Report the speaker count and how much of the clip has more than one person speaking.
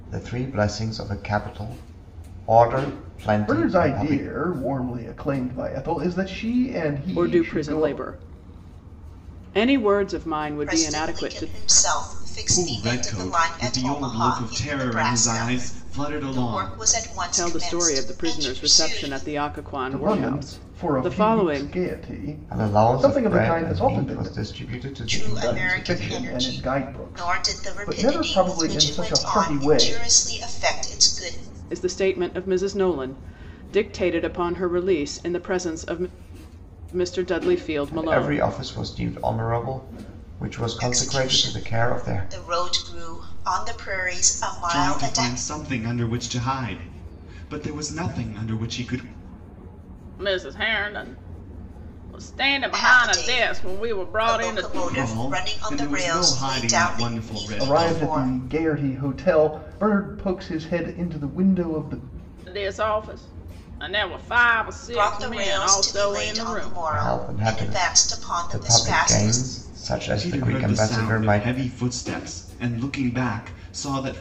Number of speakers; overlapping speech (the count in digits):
5, about 43%